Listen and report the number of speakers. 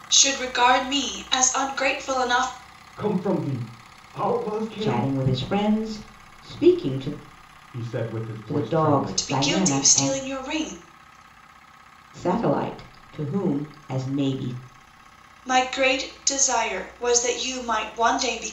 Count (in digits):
3